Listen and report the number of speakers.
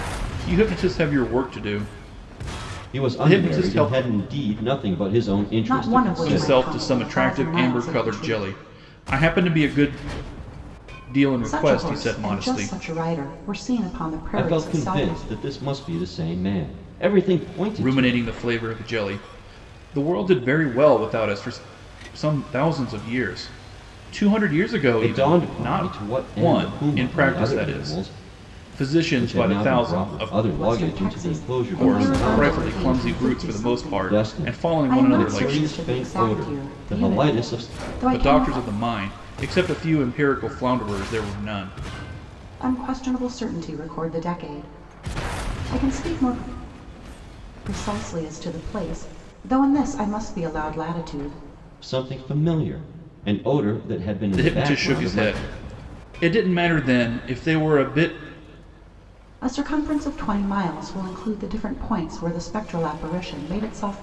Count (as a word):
three